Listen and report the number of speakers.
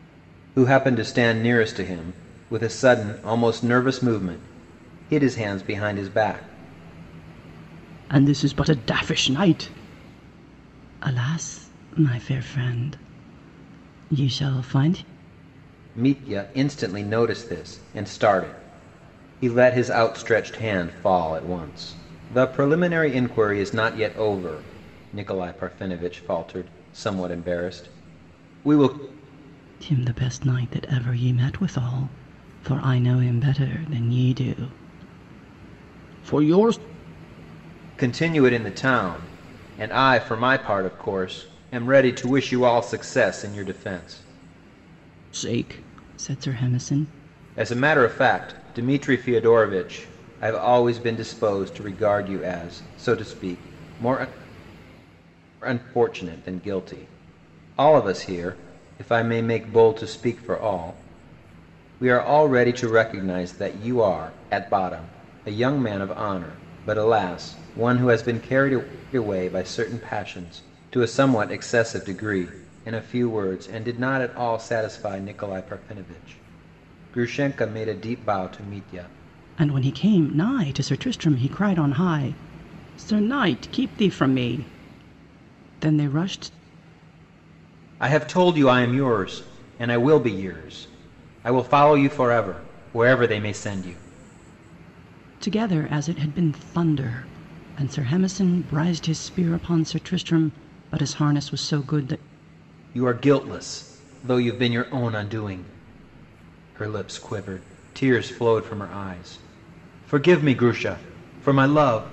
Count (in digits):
2